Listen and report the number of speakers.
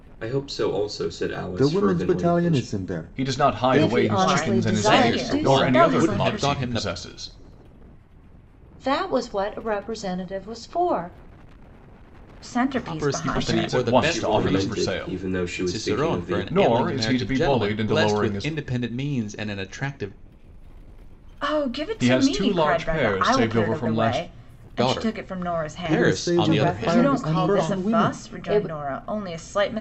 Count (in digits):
6